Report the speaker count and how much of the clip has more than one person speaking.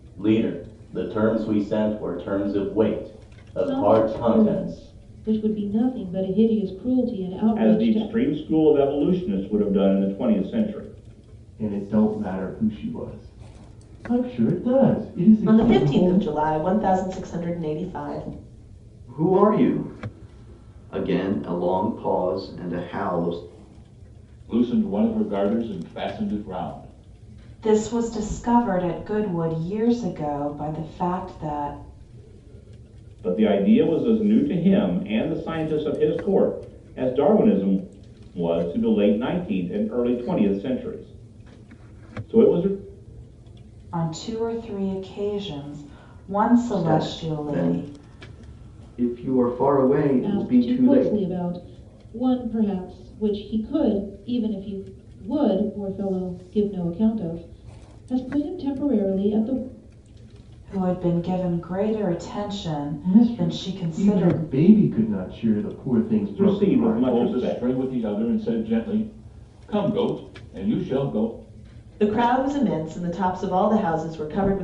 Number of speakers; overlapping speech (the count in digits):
8, about 10%